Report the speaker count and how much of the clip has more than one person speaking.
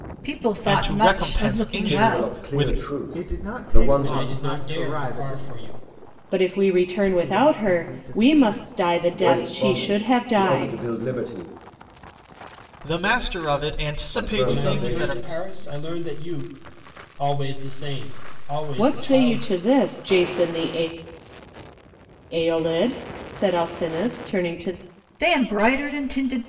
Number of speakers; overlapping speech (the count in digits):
6, about 40%